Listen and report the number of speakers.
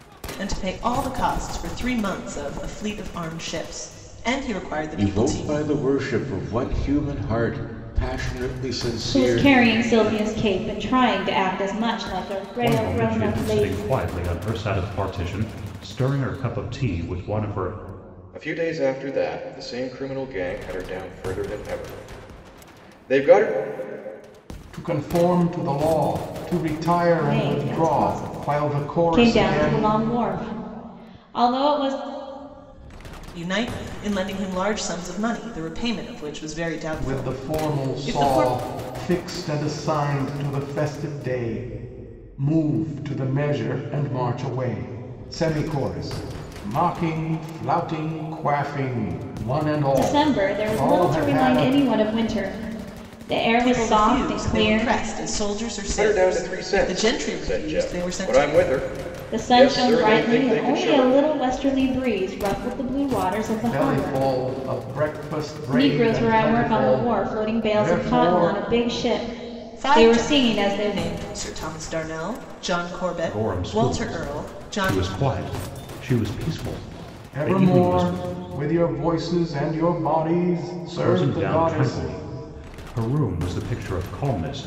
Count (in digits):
6